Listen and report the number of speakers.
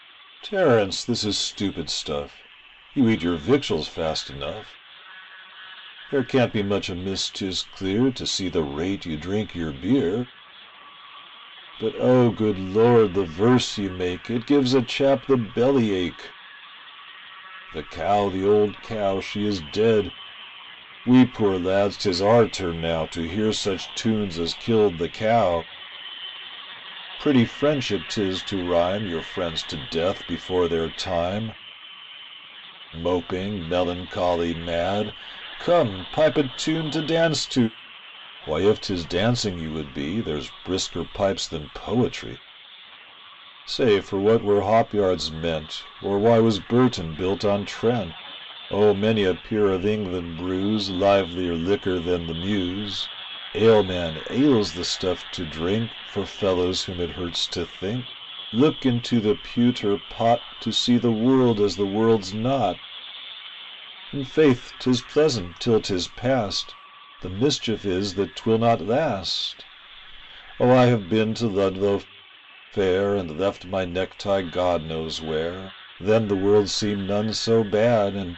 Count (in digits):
1